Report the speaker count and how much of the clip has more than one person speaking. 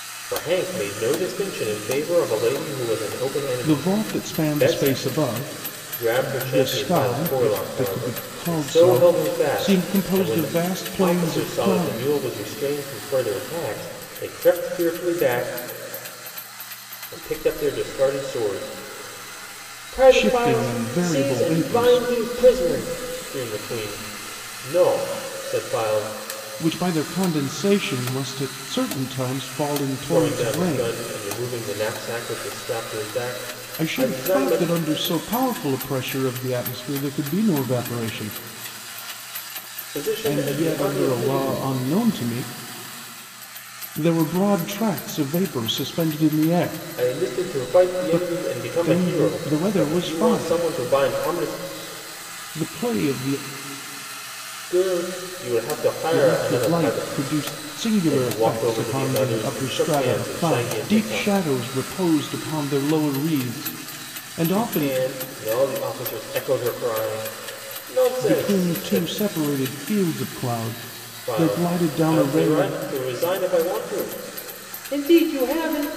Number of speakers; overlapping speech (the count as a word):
two, about 33%